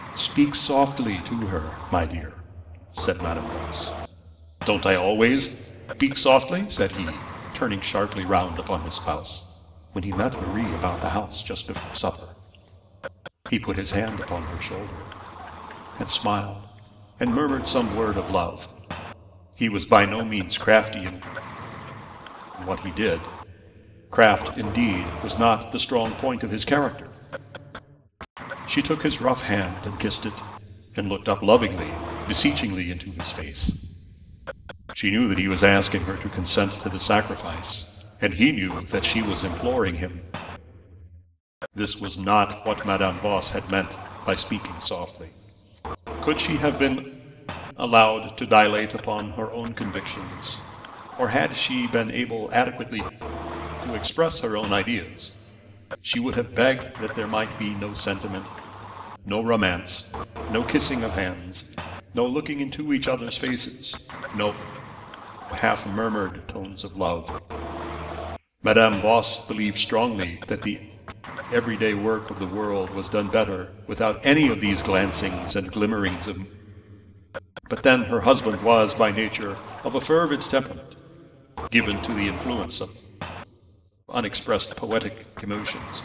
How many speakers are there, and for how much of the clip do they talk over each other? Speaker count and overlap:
1, no overlap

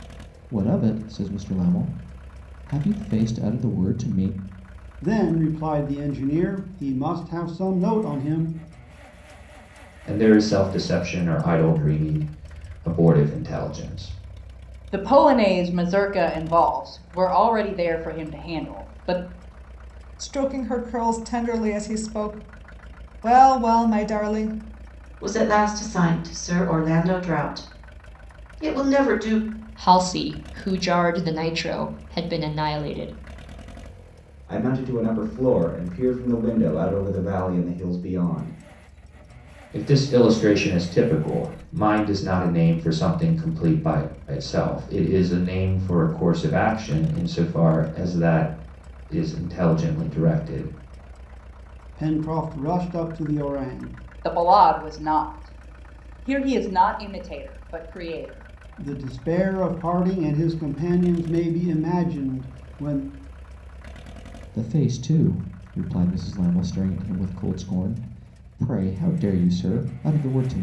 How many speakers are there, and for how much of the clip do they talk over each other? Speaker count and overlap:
8, no overlap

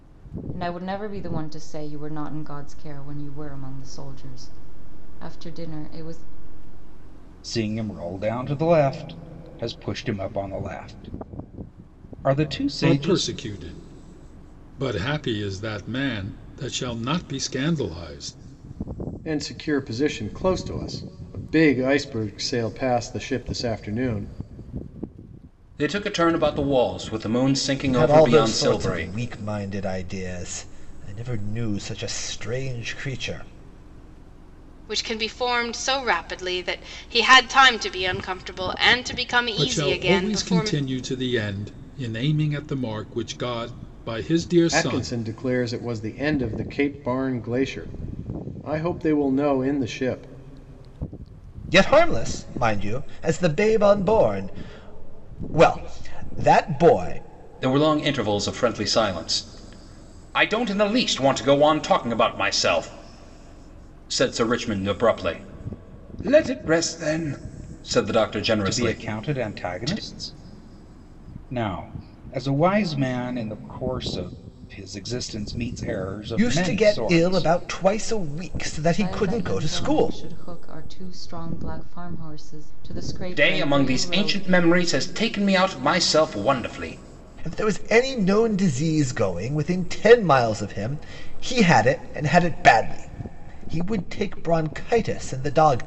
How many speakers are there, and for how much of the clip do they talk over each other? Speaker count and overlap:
7, about 9%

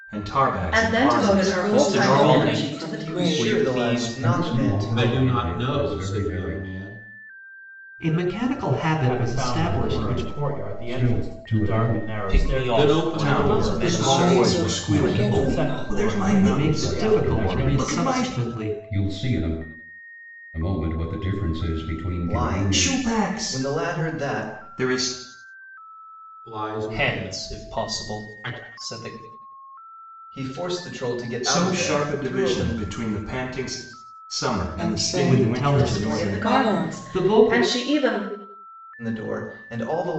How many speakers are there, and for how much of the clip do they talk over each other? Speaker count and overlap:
9, about 59%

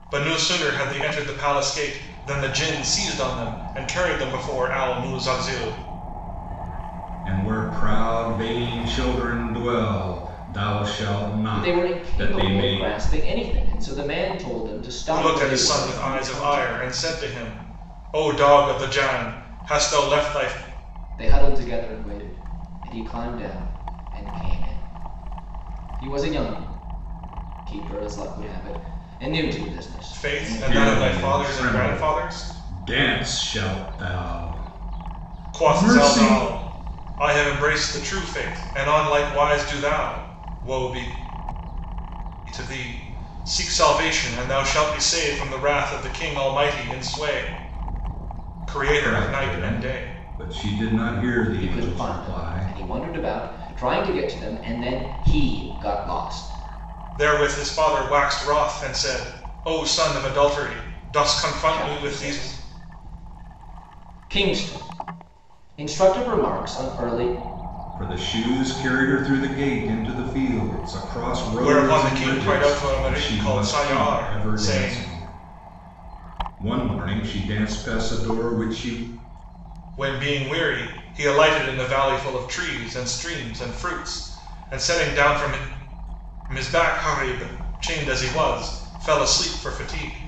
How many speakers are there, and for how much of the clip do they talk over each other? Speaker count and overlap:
3, about 15%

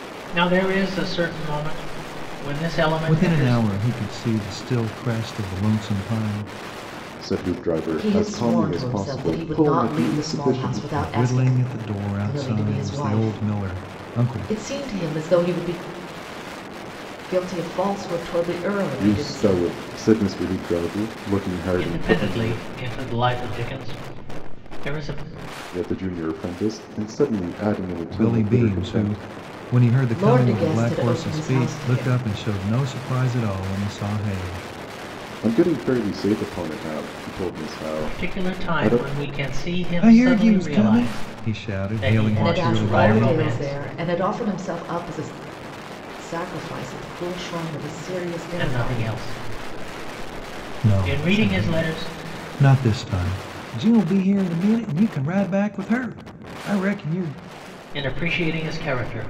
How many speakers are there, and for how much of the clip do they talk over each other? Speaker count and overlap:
4, about 29%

